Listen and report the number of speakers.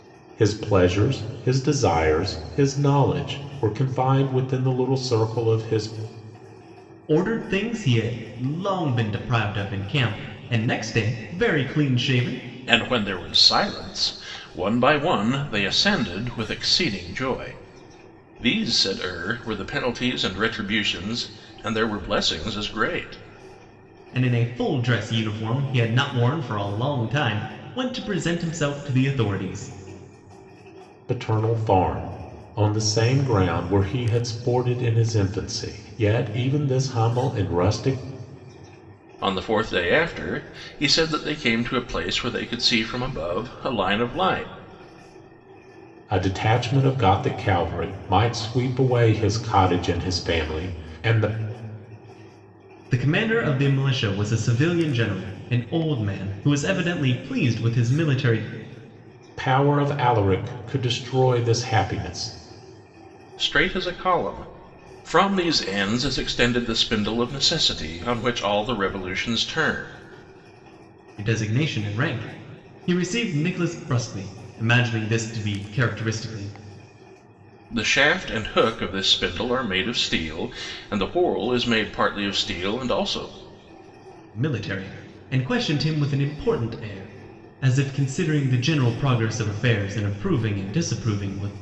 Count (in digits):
3